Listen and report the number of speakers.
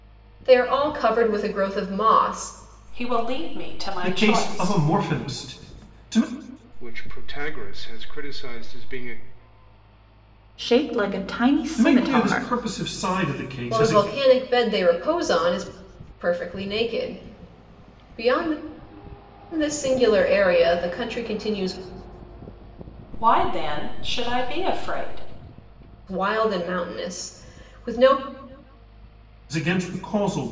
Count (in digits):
5